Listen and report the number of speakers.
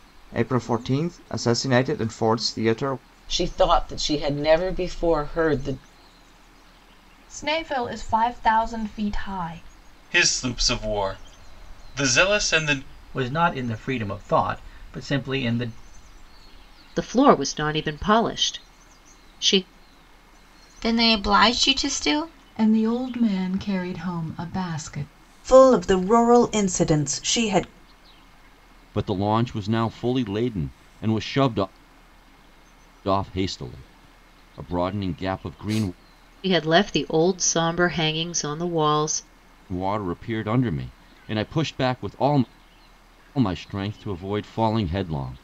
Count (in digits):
10